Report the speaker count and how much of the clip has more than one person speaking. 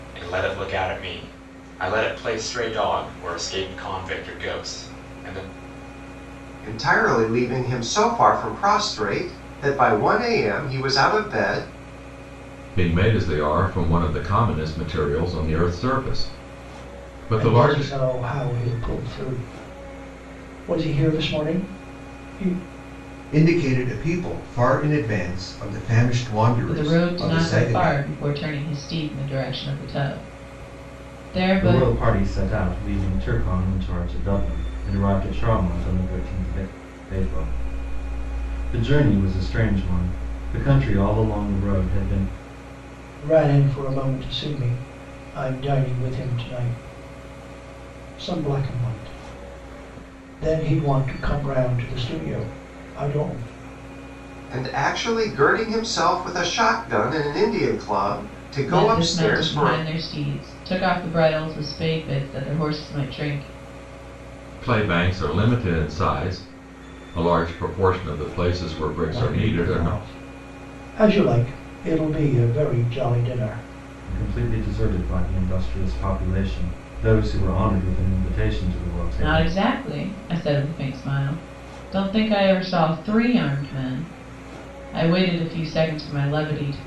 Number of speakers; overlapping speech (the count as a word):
seven, about 6%